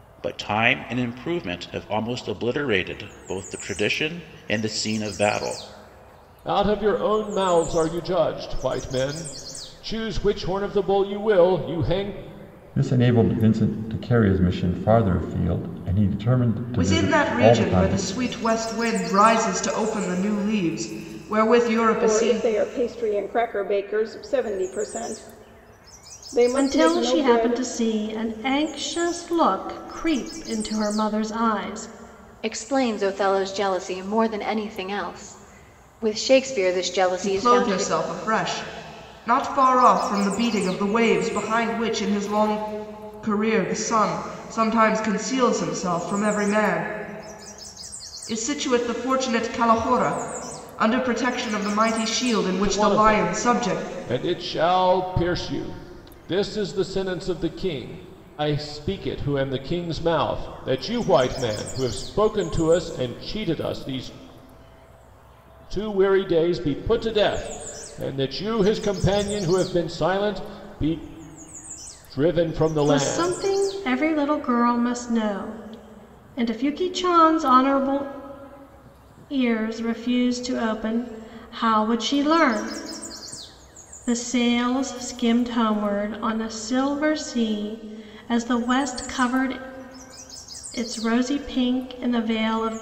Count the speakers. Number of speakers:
seven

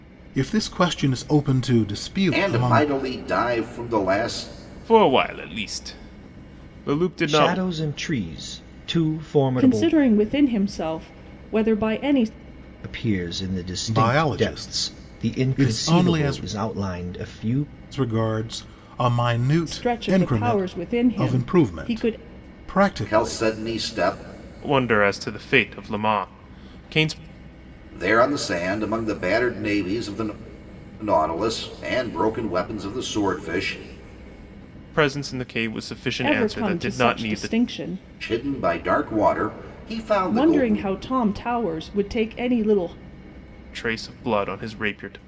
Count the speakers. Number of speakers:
five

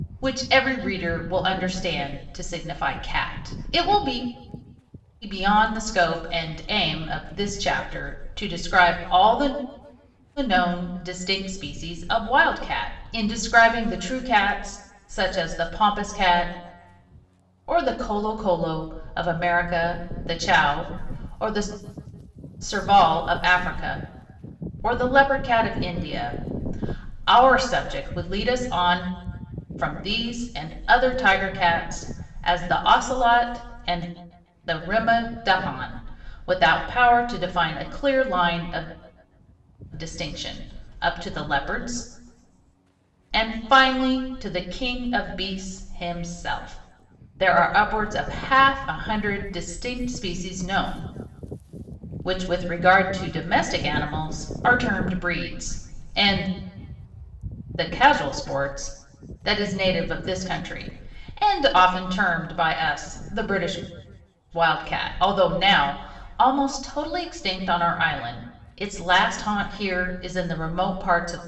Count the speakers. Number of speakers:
one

